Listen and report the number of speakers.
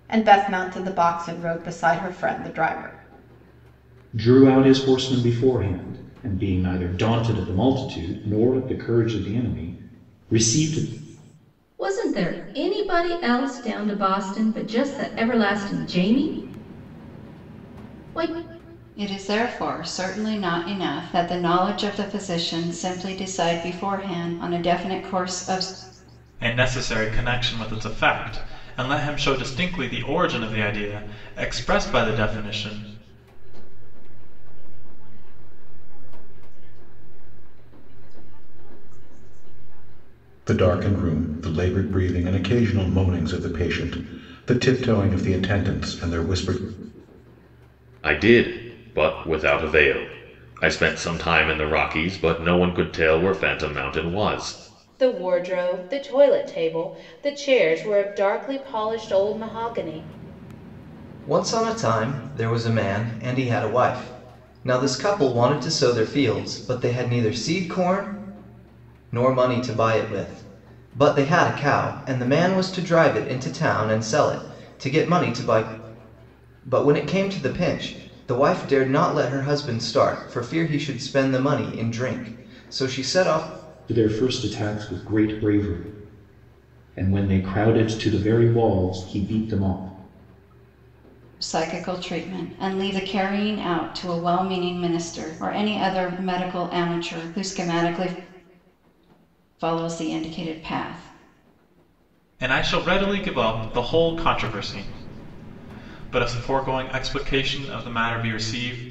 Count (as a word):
ten